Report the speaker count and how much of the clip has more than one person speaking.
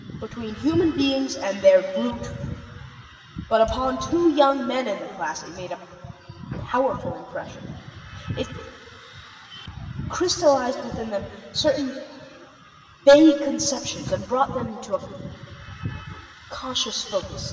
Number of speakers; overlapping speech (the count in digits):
1, no overlap